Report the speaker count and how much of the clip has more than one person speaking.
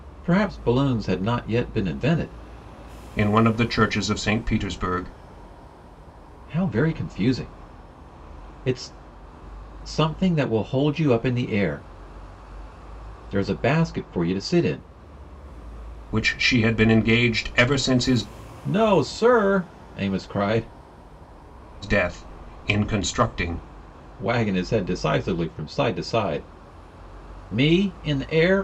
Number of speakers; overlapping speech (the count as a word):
two, no overlap